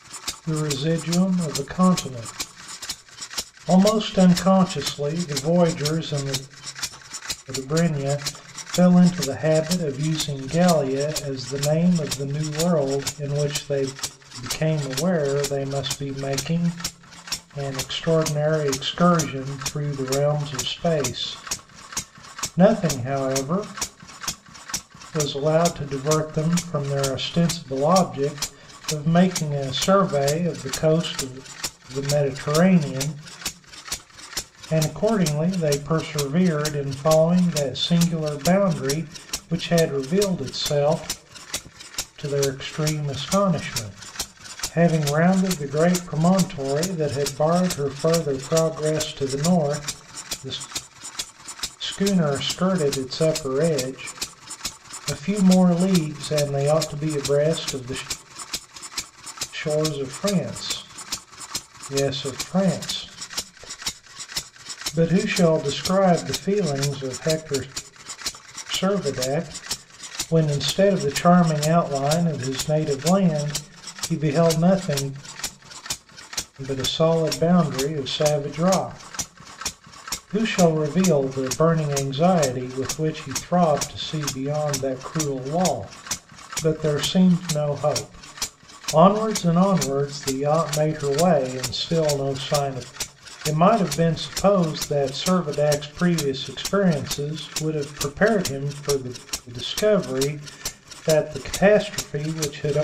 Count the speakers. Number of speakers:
1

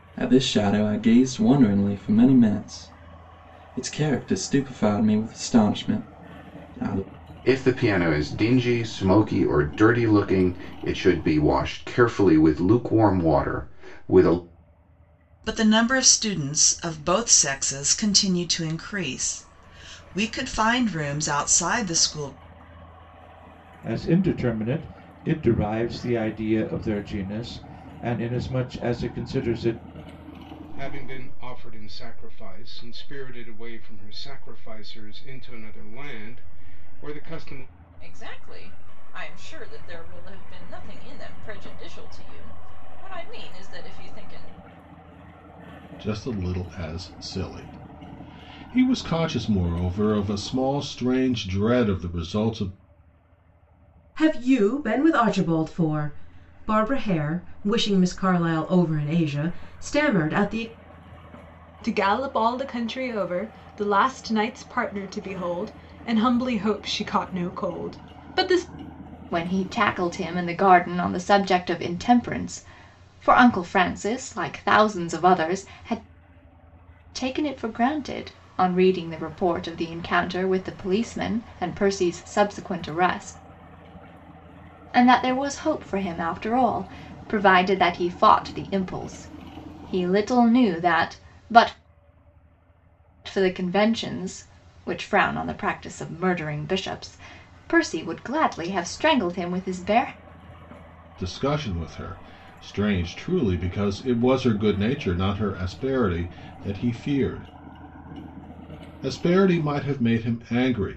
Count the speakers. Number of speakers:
10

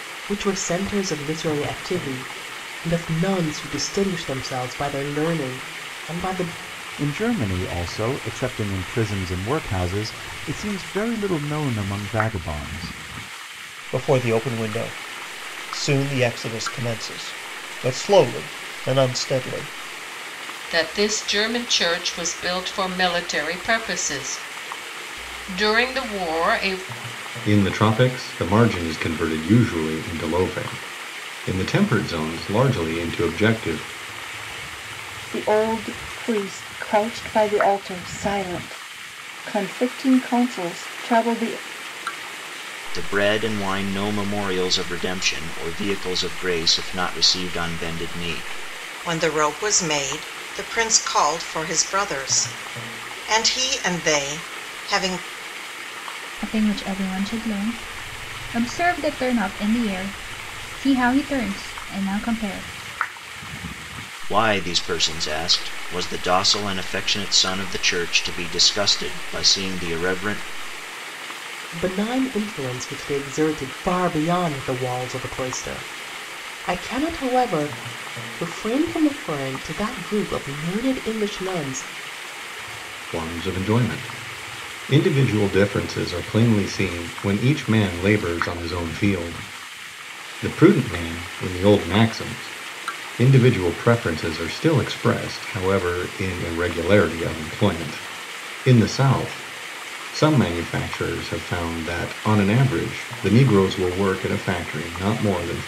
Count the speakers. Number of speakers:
9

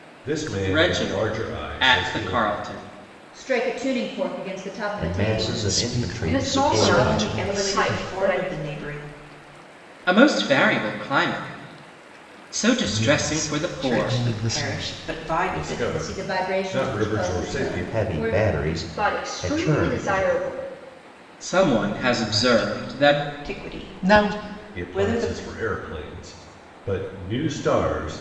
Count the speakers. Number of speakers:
7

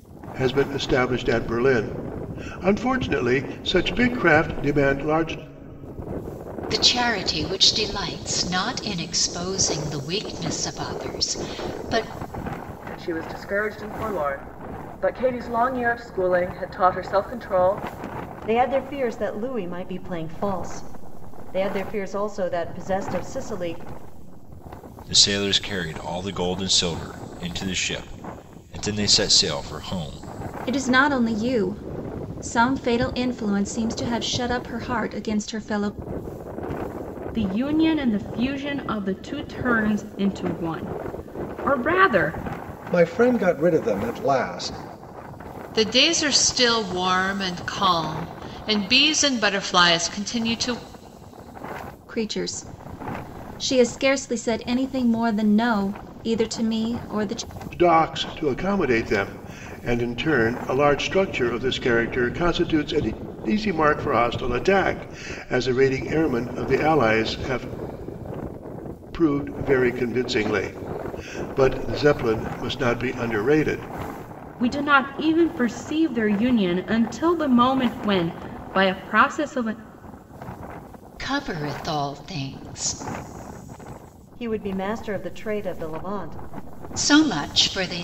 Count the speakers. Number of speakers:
9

